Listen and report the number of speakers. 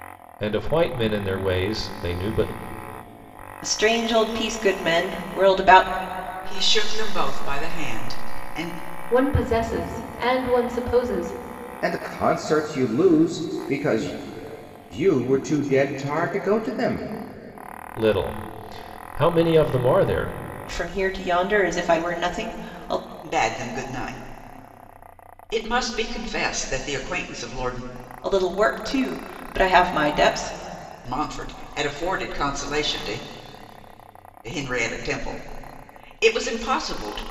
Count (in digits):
5